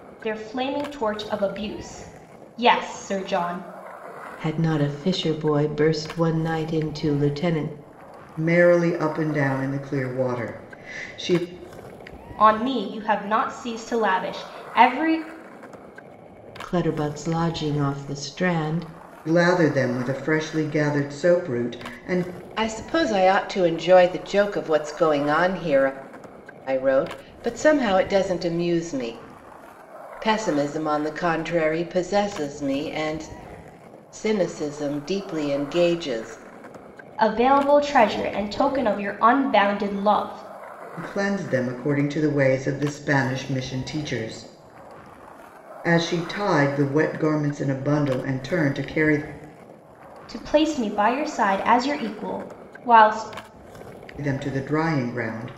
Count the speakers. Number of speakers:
3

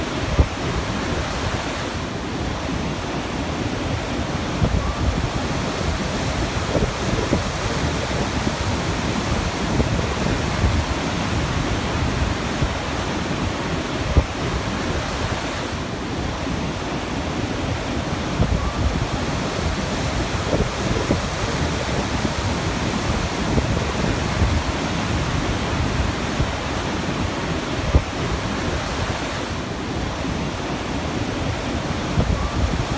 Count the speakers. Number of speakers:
0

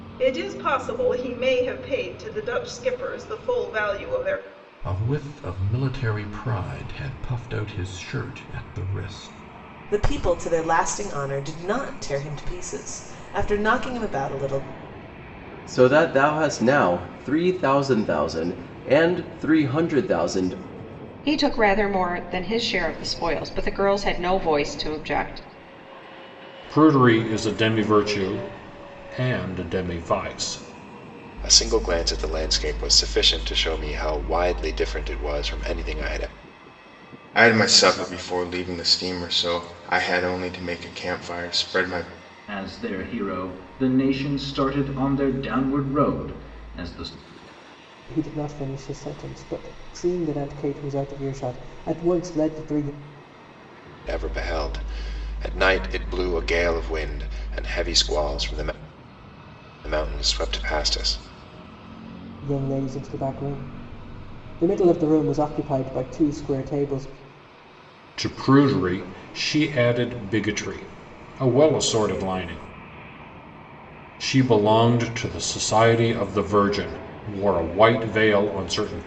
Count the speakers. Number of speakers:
10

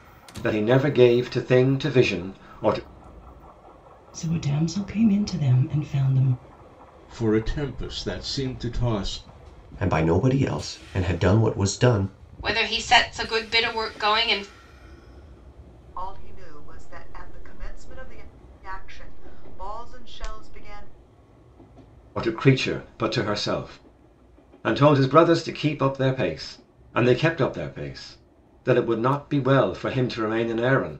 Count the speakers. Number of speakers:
6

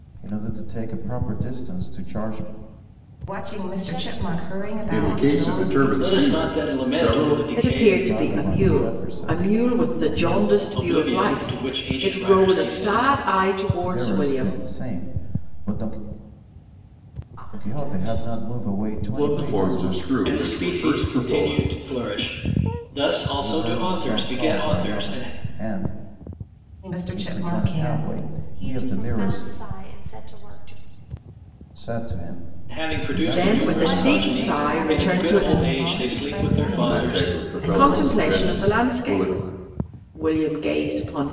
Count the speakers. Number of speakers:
6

